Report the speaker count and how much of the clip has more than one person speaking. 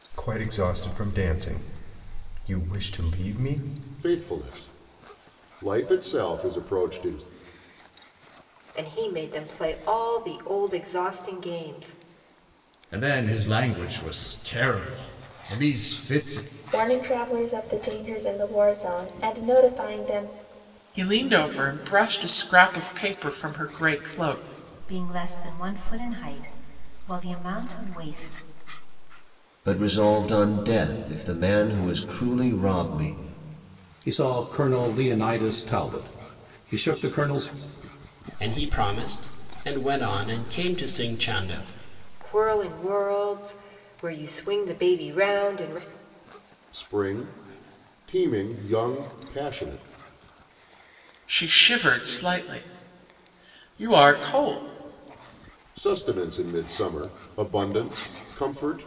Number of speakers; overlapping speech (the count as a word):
ten, no overlap